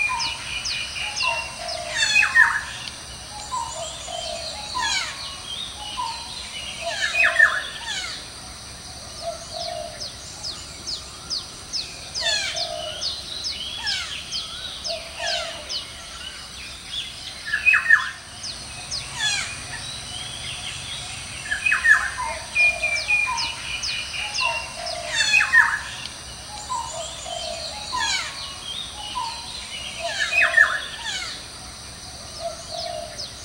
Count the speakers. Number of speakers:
0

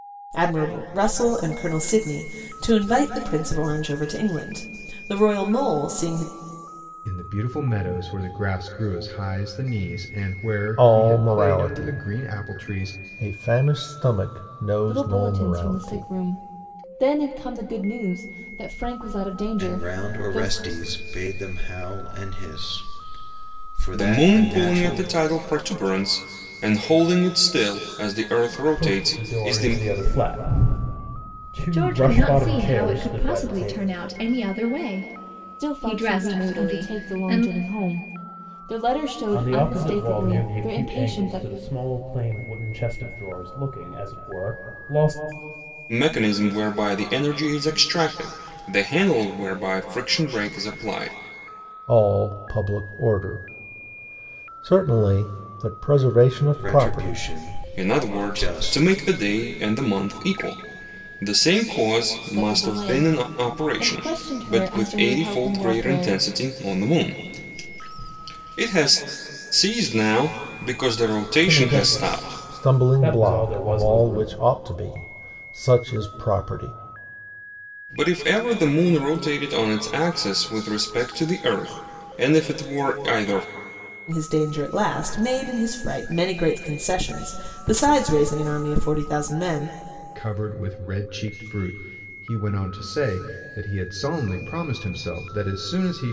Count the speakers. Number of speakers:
8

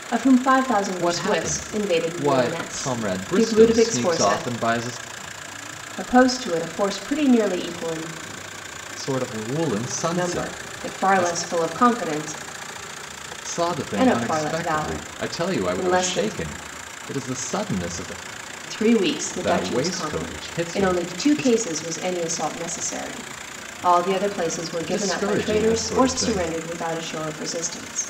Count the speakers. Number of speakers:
2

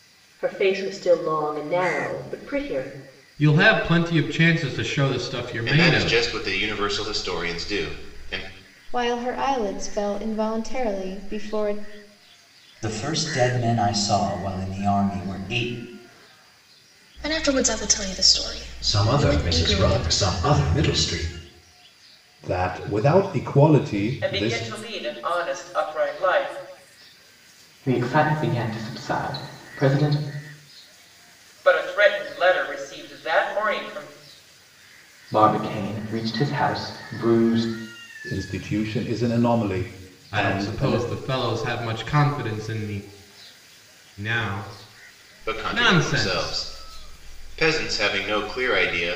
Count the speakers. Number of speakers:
10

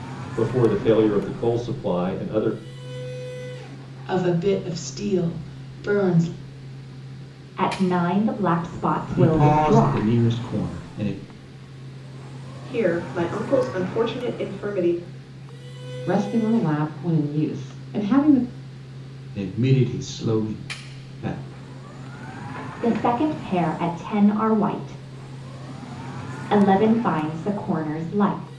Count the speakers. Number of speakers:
6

